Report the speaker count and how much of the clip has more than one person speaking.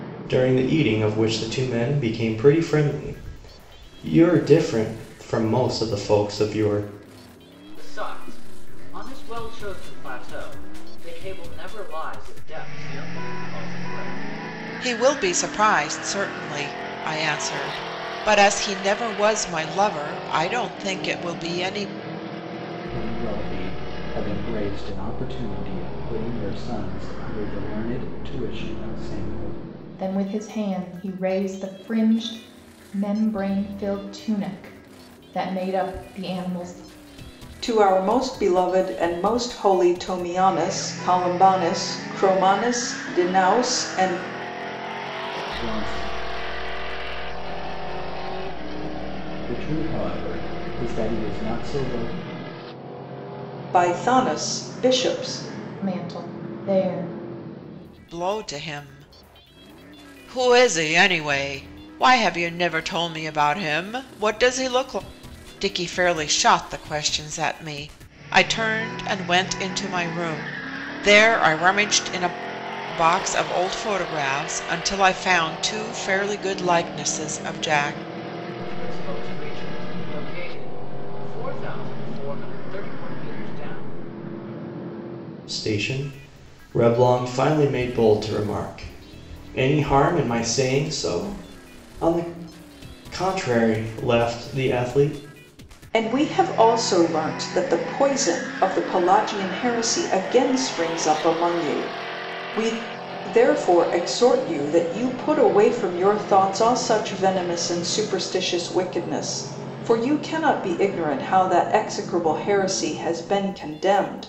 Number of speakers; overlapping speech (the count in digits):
6, no overlap